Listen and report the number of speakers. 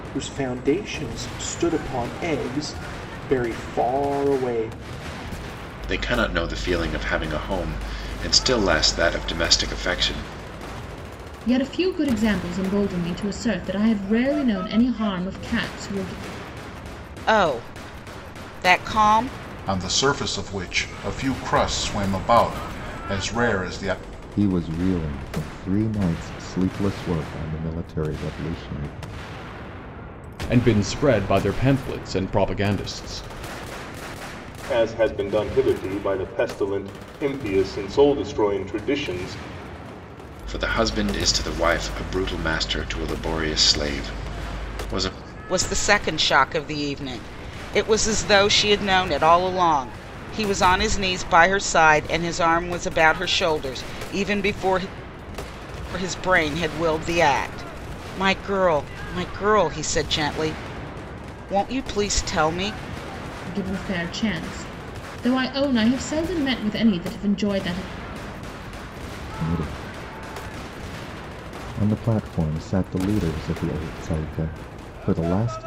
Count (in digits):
8